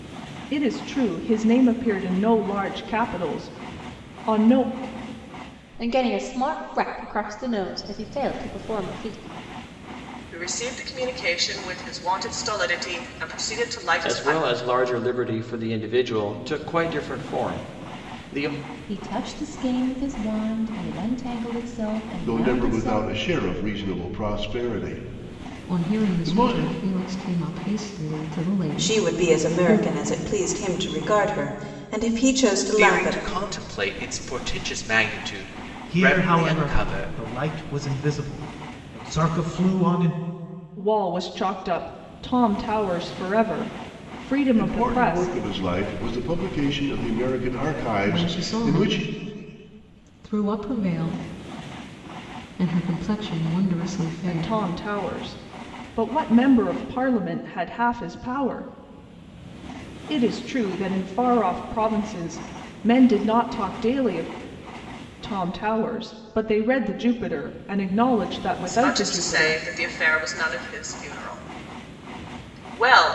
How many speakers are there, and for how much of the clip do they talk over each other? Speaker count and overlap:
ten, about 12%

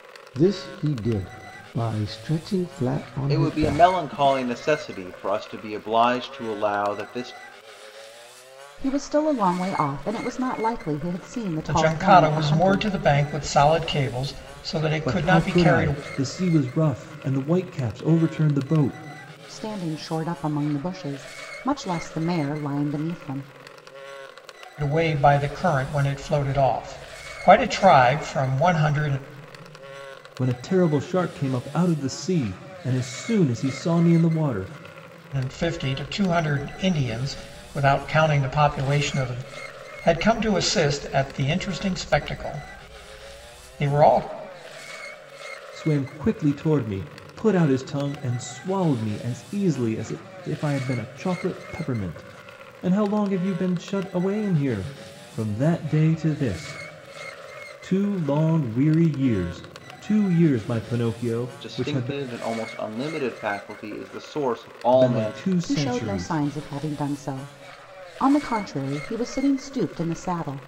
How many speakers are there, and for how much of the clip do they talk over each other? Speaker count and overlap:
five, about 7%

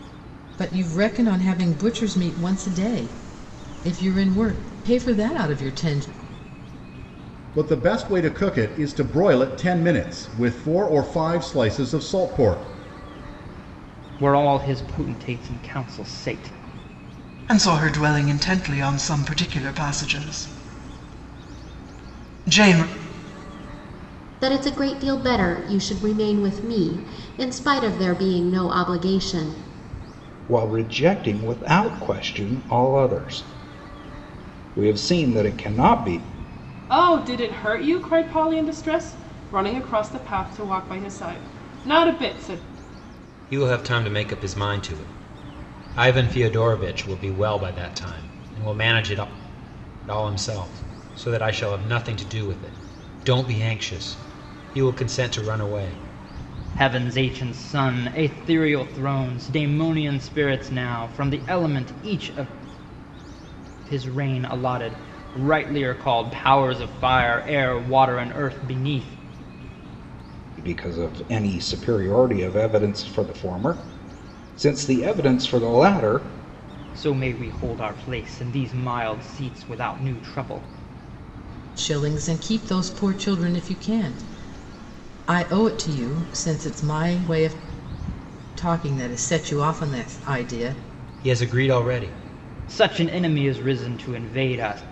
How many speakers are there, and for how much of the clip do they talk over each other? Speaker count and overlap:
eight, no overlap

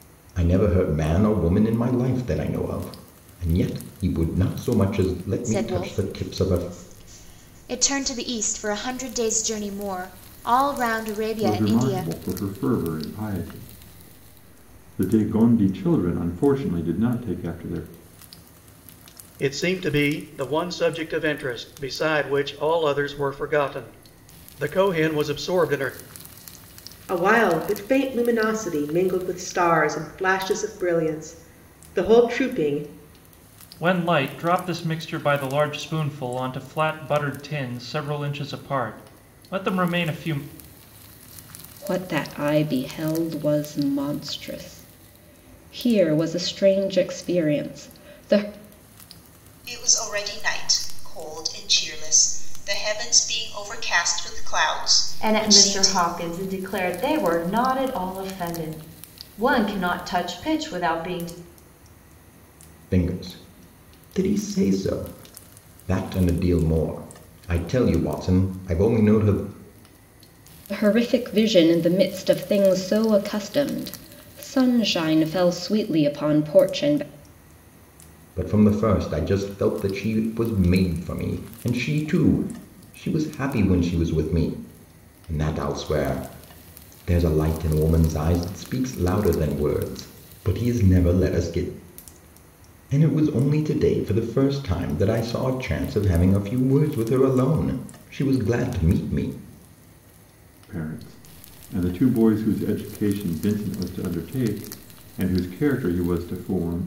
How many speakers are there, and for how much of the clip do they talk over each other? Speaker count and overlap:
nine, about 3%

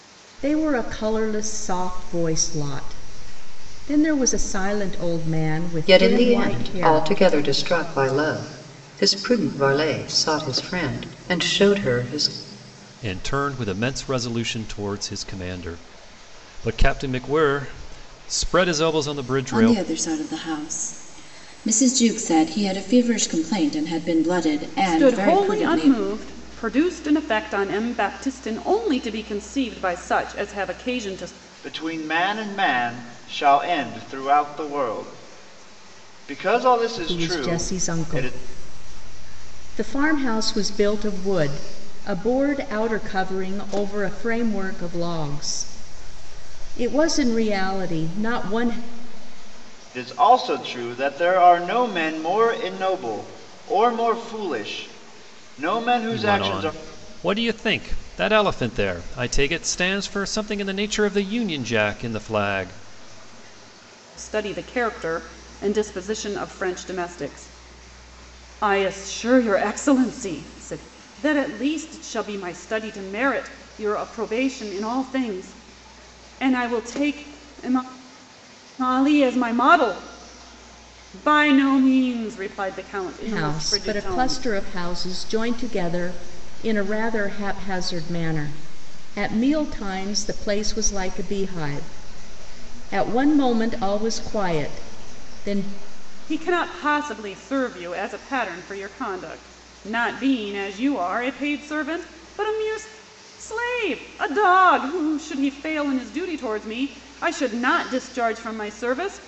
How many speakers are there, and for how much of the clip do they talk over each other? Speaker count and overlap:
six, about 6%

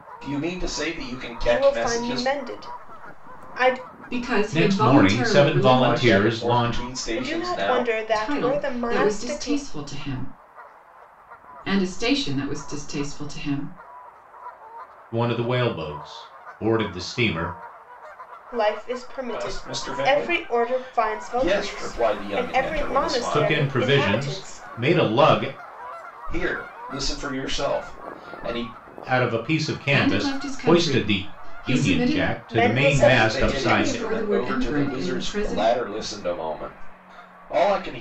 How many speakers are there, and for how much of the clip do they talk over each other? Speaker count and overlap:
four, about 42%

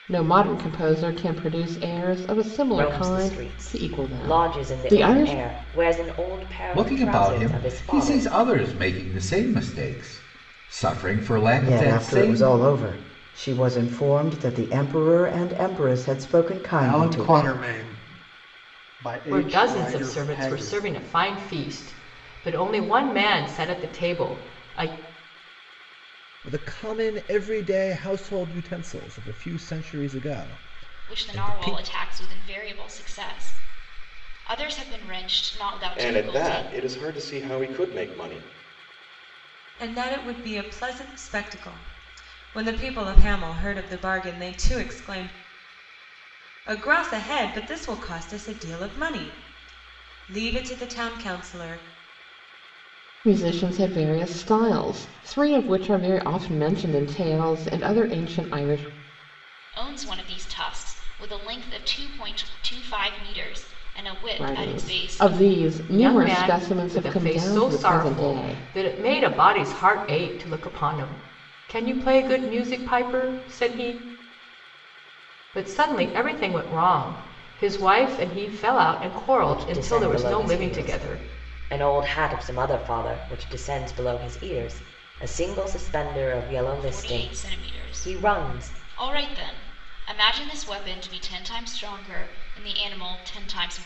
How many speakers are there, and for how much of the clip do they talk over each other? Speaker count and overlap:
ten, about 18%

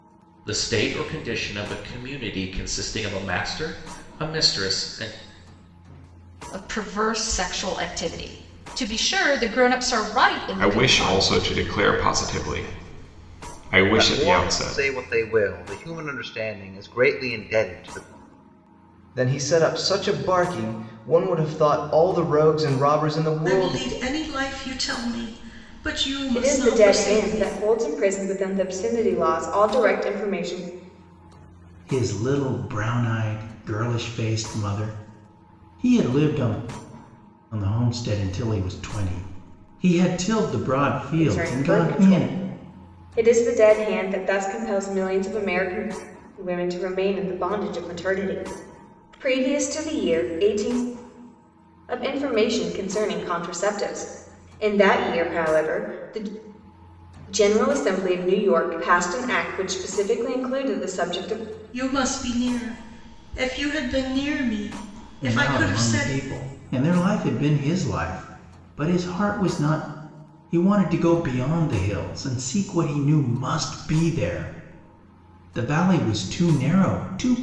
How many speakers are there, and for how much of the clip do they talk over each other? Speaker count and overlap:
eight, about 7%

